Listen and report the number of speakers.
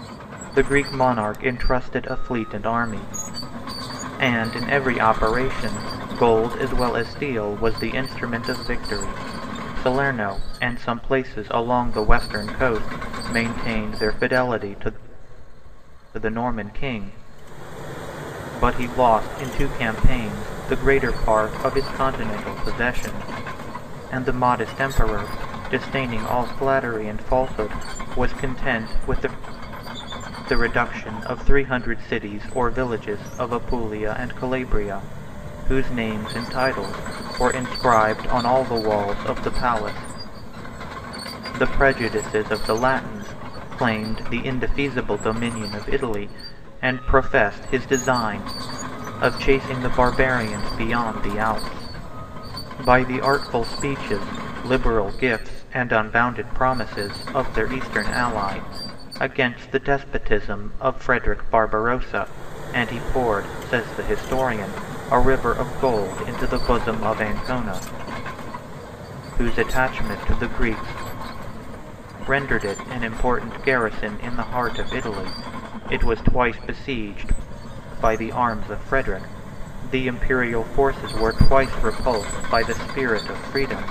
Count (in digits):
1